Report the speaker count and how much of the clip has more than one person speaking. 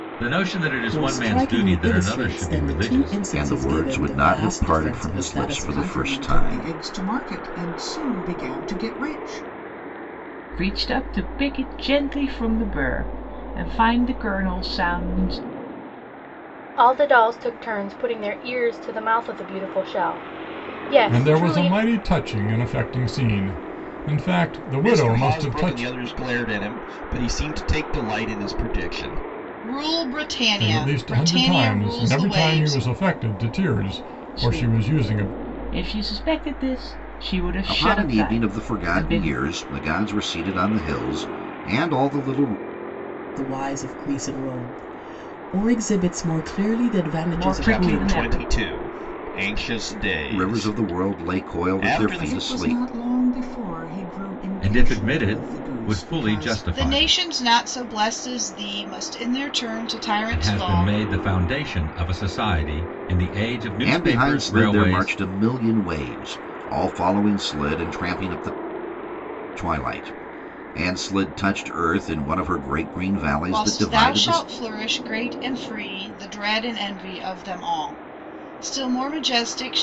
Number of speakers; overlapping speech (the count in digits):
9, about 28%